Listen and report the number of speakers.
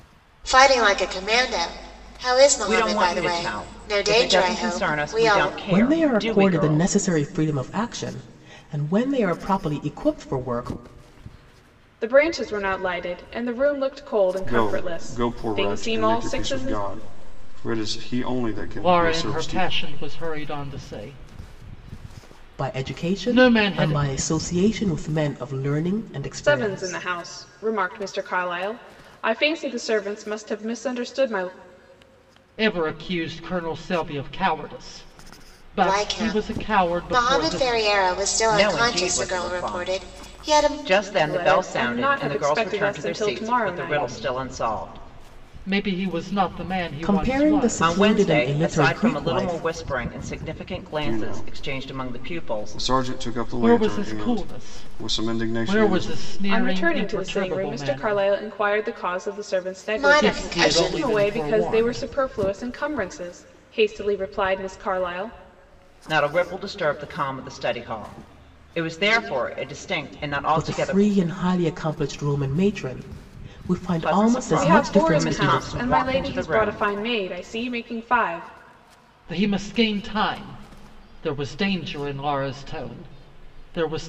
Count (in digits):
6